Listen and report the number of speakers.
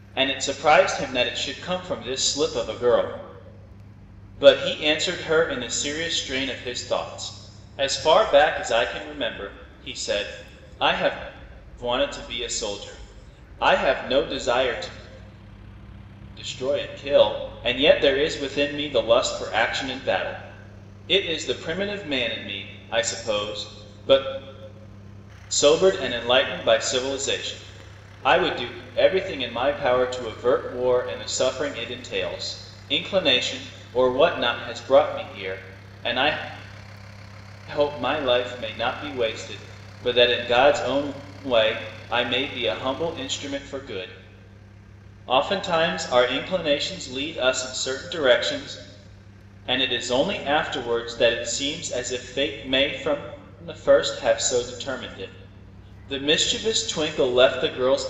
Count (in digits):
1